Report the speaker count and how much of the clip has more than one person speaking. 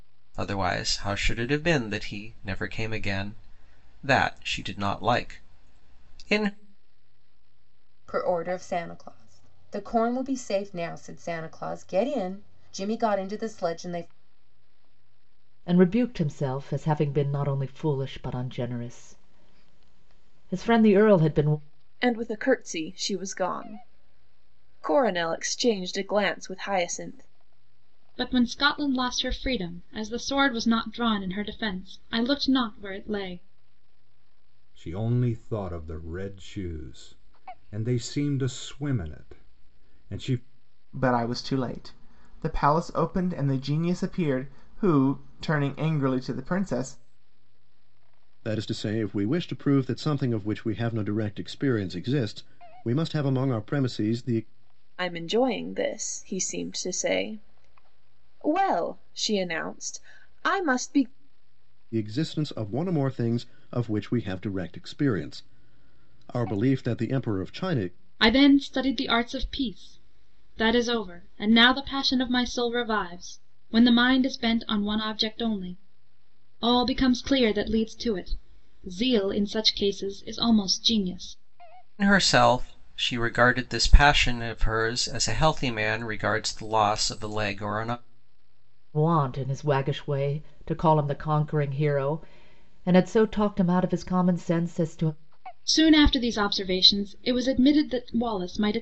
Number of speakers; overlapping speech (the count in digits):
8, no overlap